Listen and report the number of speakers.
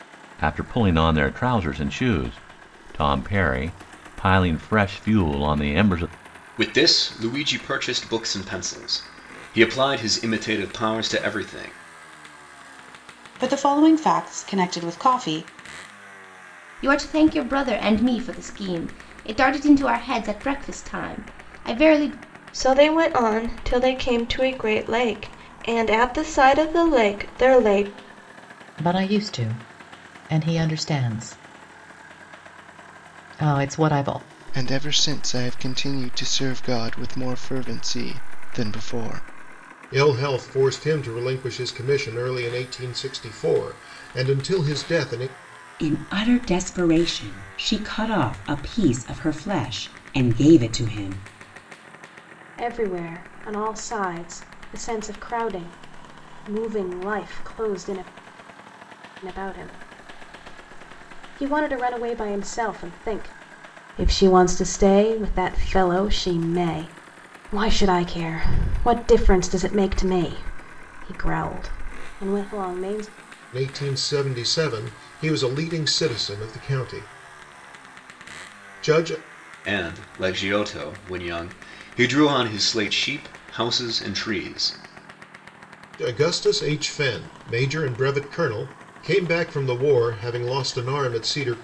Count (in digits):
10